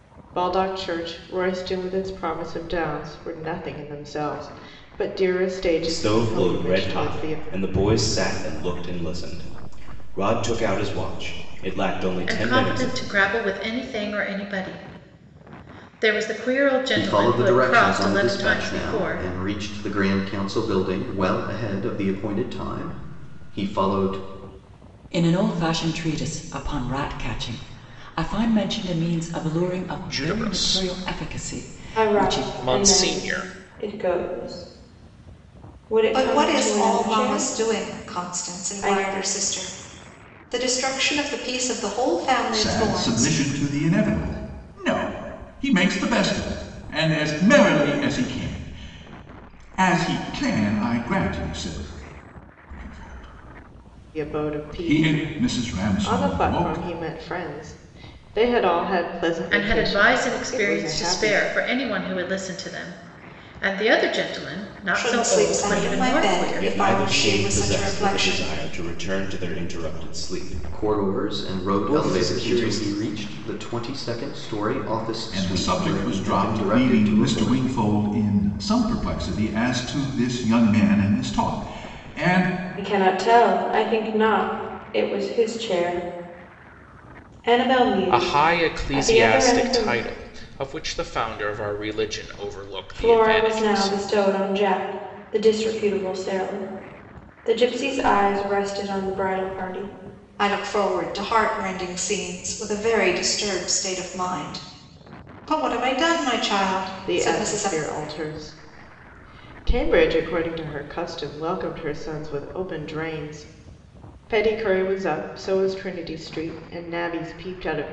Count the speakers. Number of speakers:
9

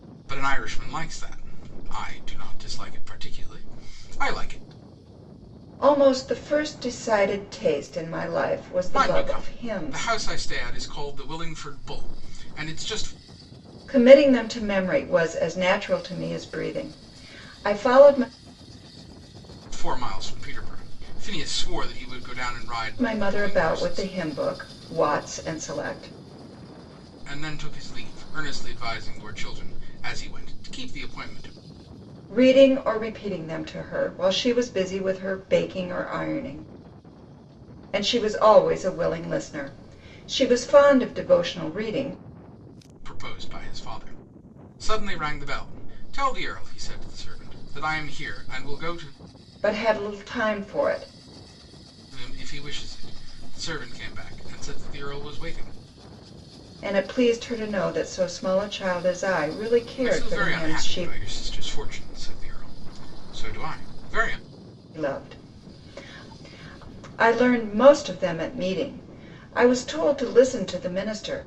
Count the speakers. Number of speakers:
2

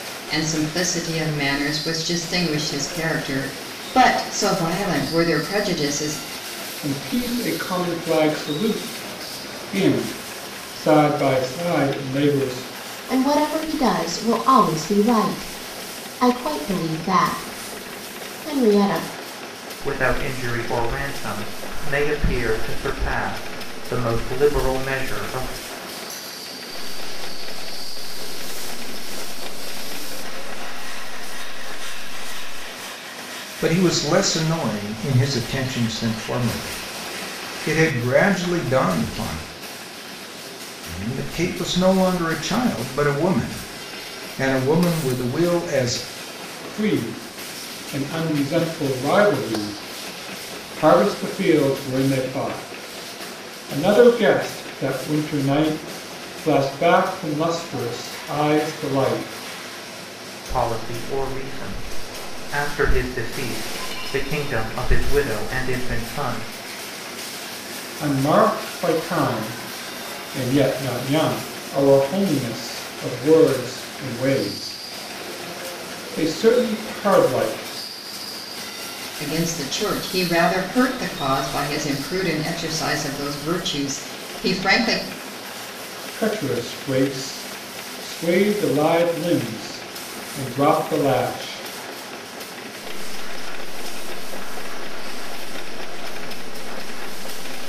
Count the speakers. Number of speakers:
6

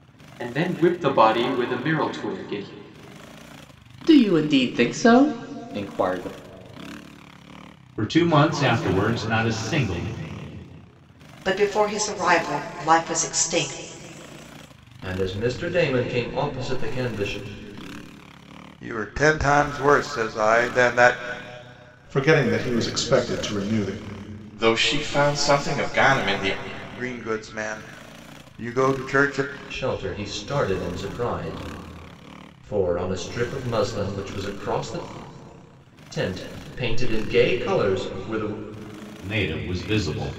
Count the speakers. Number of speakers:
8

